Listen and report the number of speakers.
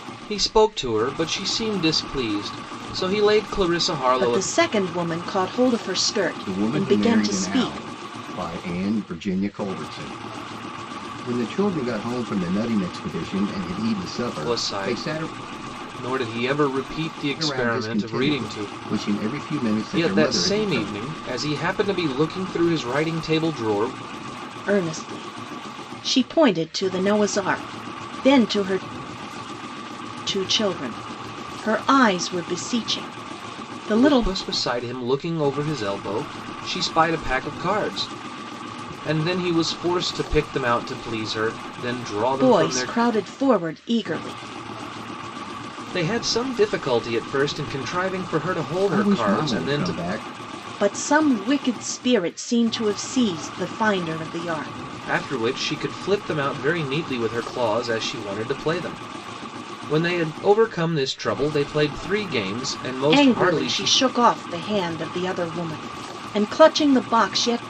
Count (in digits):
3